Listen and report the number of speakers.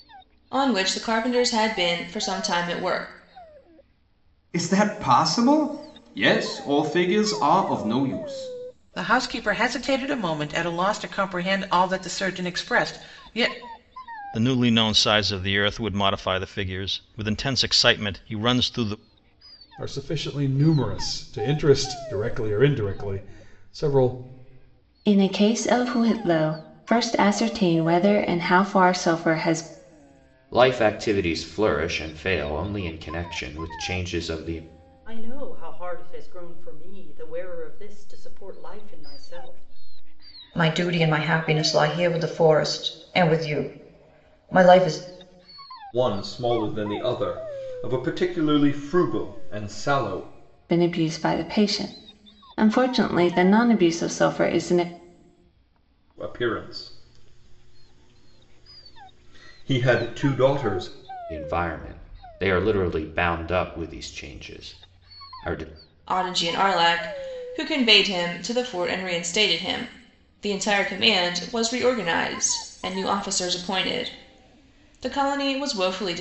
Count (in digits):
10